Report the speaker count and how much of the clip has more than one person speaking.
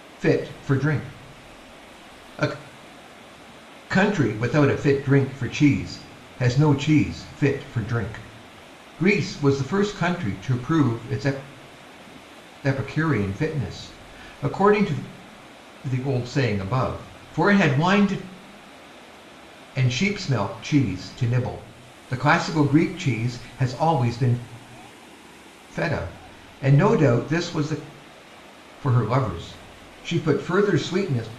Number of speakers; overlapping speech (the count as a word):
one, no overlap